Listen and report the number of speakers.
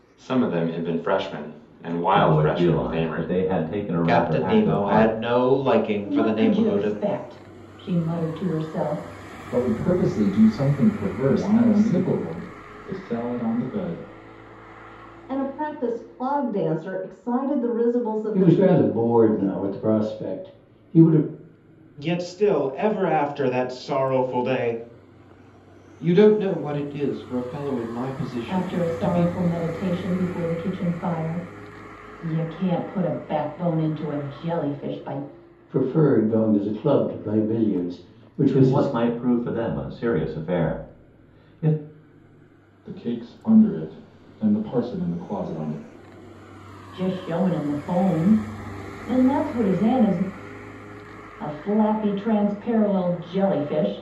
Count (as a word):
ten